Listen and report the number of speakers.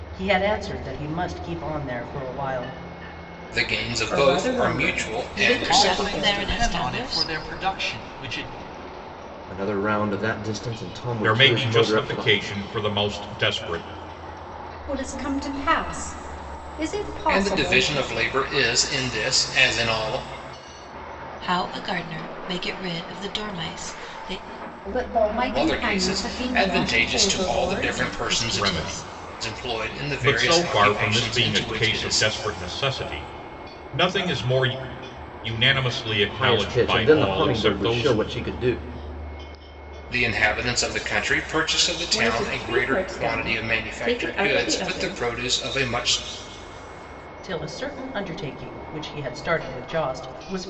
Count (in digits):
8